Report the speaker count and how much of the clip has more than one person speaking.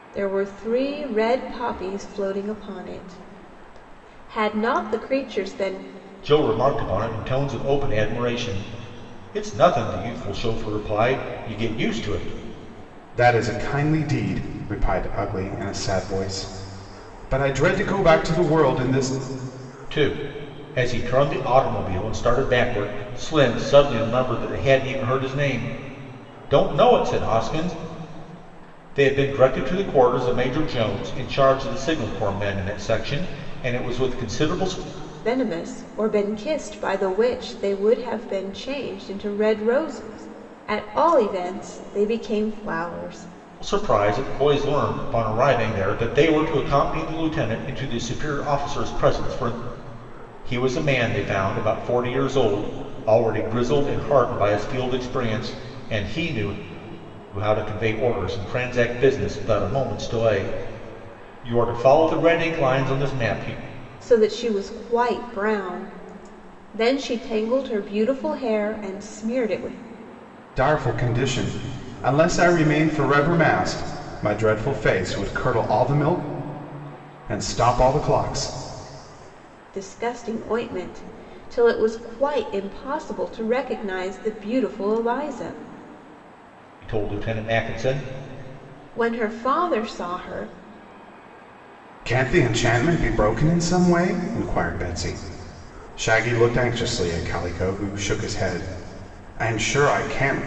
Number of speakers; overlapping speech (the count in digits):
3, no overlap